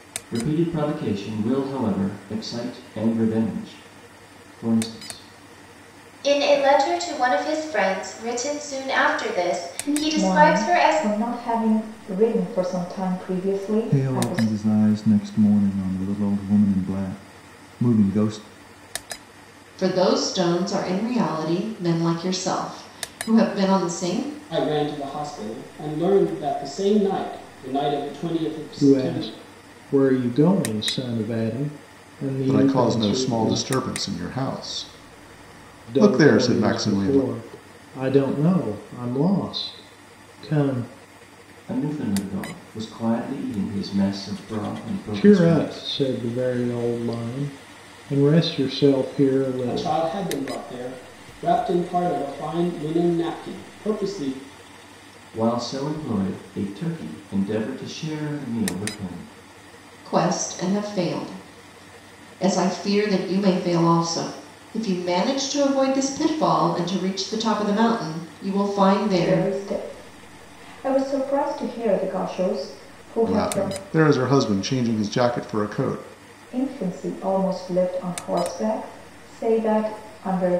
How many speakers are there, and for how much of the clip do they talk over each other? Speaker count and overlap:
8, about 9%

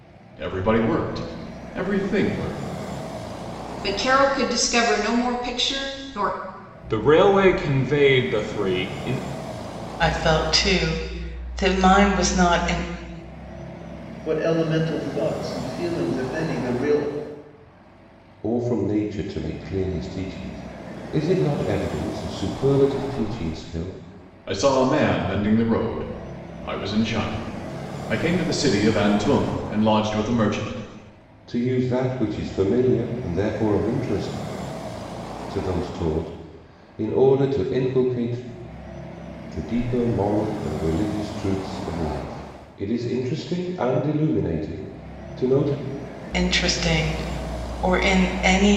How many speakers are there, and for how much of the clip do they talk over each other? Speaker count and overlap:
6, no overlap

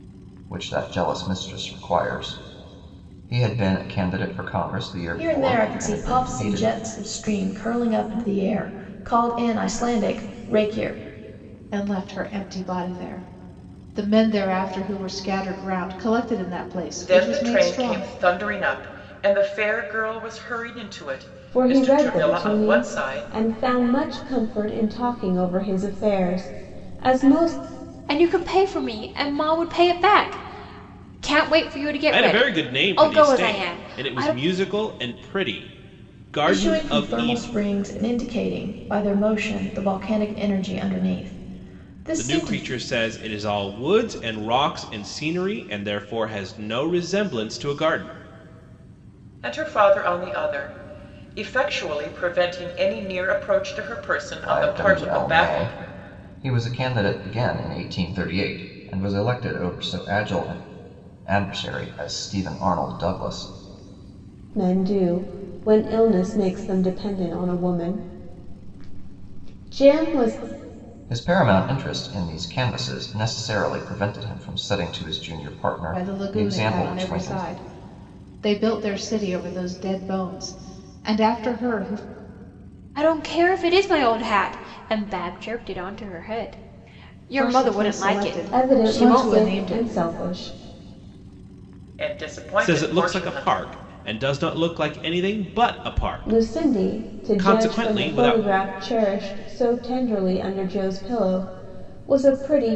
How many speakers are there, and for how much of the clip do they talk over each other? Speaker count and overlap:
7, about 17%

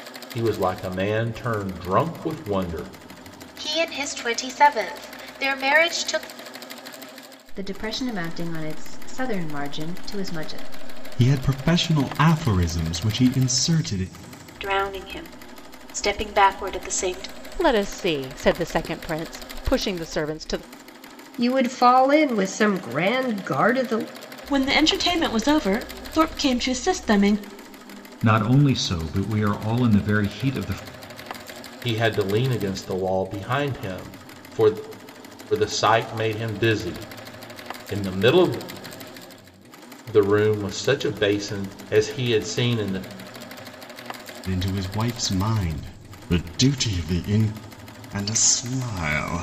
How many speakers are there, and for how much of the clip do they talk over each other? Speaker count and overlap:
9, no overlap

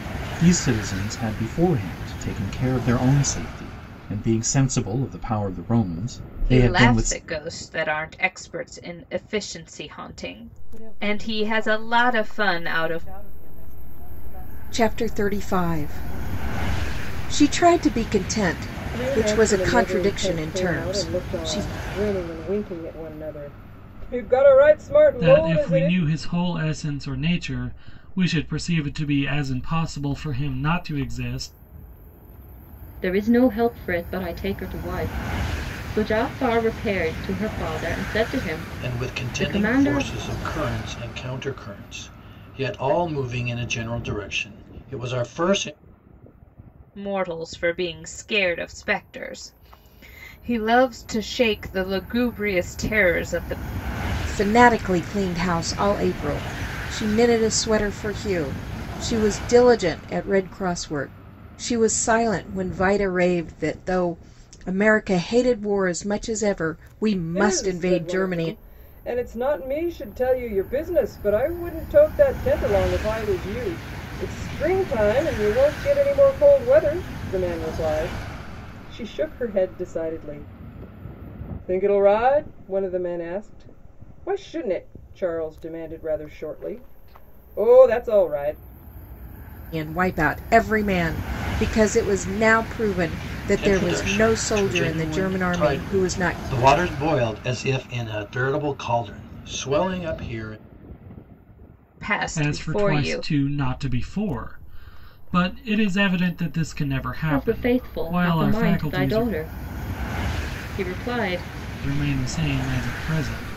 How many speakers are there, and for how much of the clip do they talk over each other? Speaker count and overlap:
8, about 16%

